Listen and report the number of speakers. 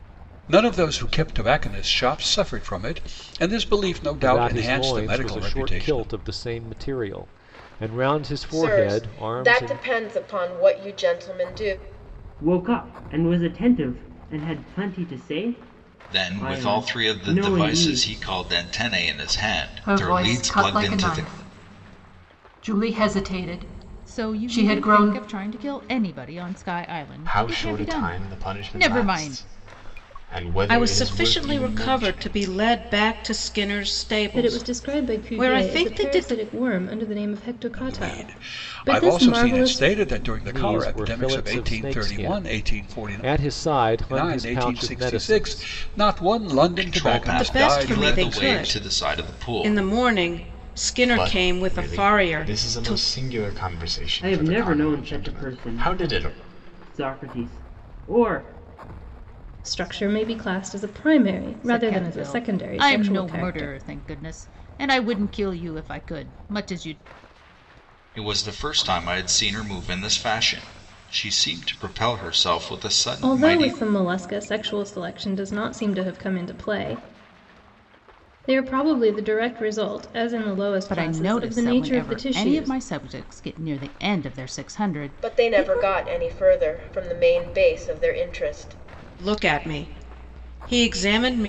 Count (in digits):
10